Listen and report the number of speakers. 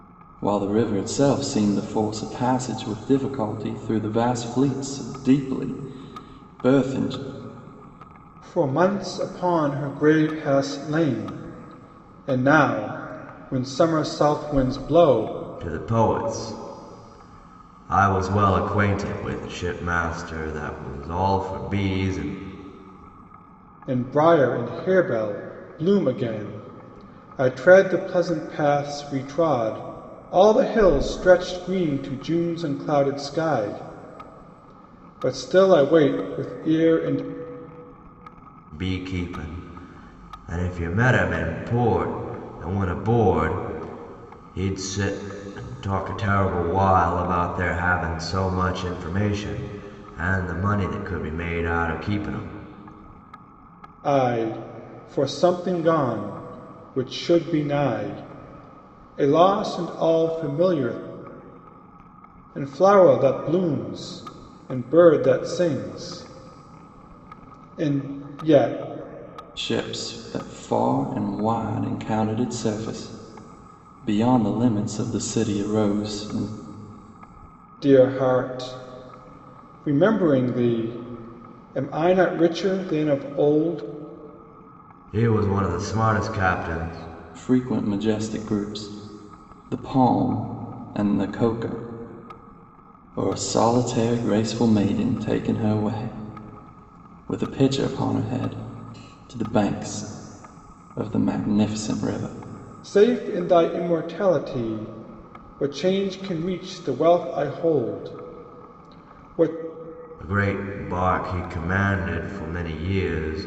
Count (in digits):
3